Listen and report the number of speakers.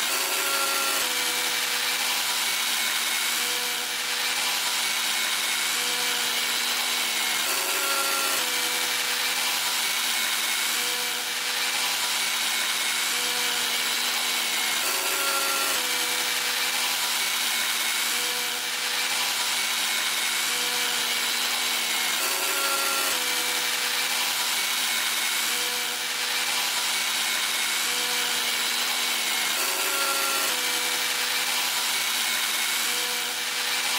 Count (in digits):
0